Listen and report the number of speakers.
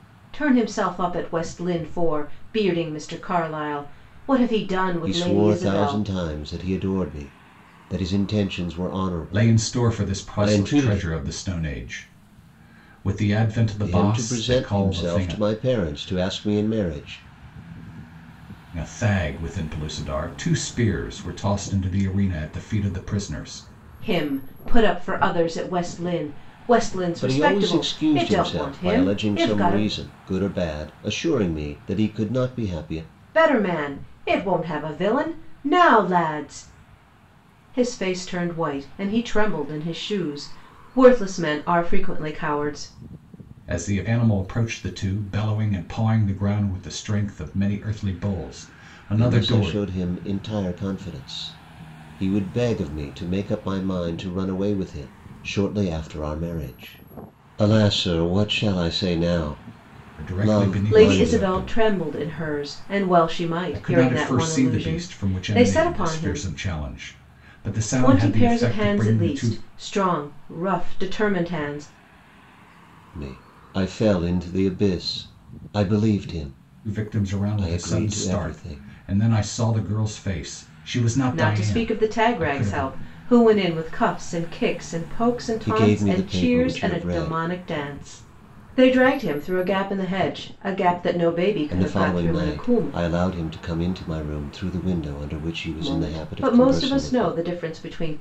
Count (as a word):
three